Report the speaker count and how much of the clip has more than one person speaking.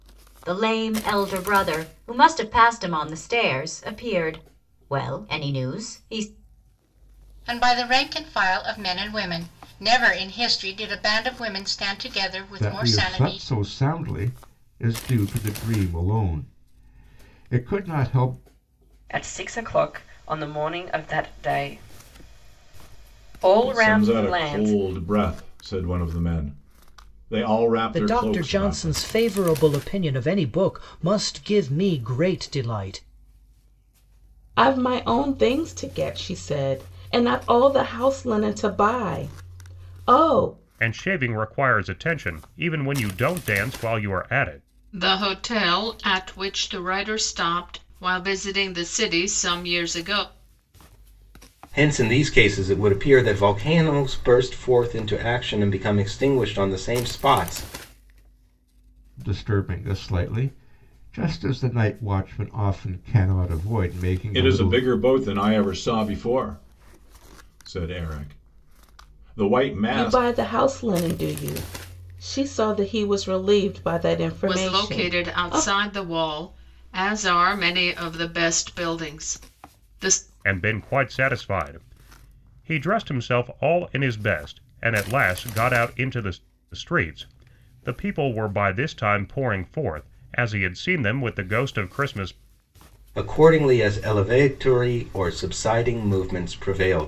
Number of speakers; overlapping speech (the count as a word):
ten, about 6%